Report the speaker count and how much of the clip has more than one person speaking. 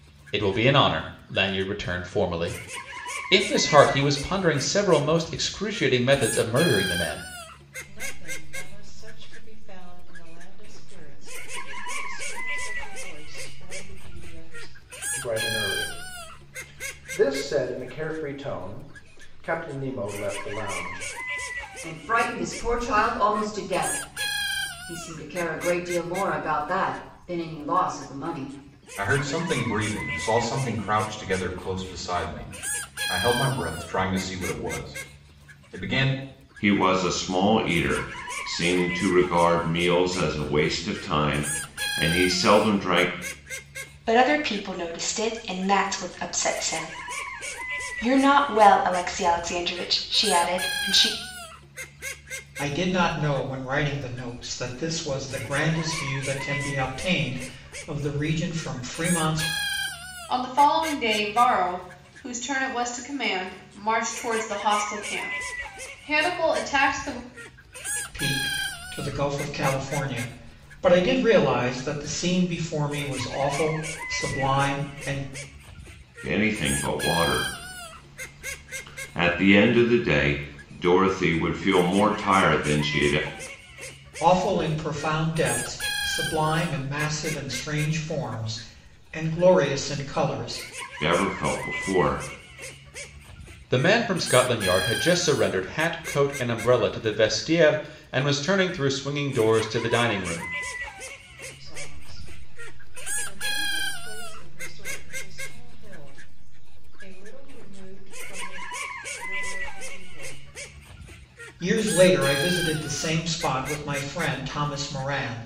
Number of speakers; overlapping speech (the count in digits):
9, no overlap